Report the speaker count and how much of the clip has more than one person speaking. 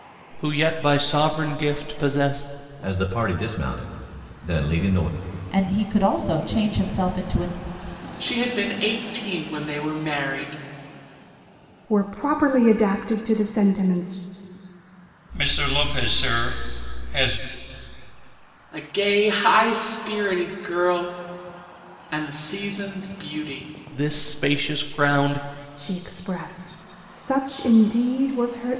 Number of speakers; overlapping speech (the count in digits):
6, no overlap